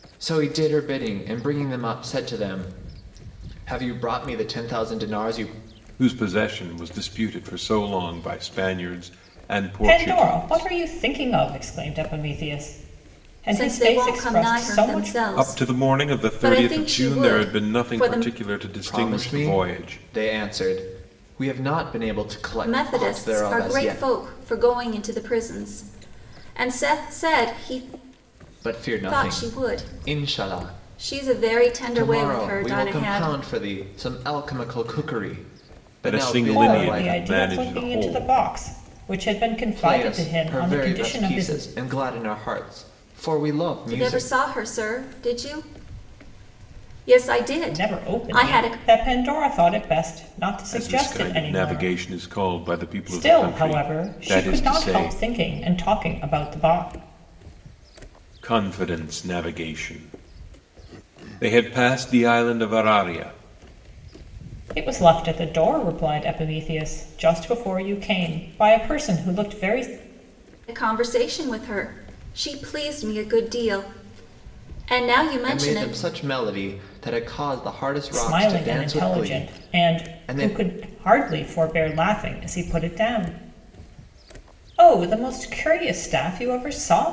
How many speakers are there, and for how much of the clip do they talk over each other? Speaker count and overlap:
4, about 28%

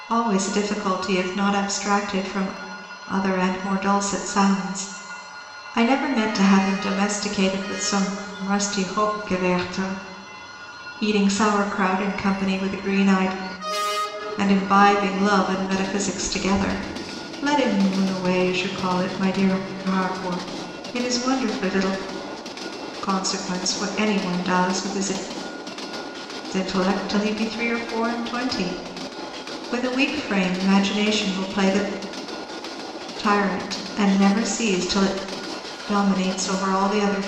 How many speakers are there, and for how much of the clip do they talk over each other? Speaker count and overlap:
1, no overlap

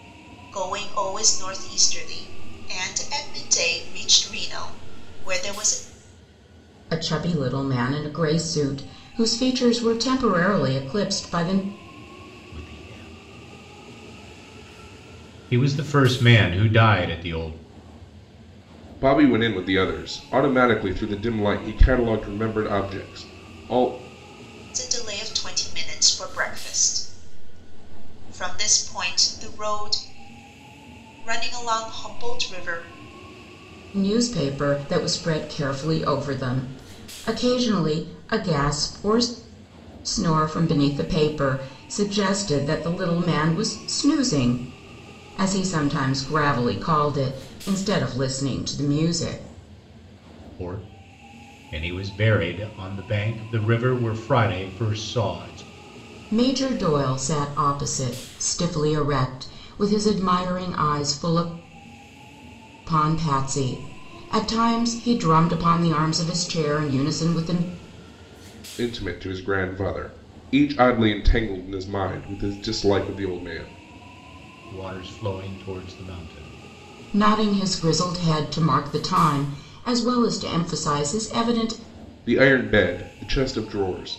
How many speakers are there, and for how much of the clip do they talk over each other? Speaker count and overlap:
4, no overlap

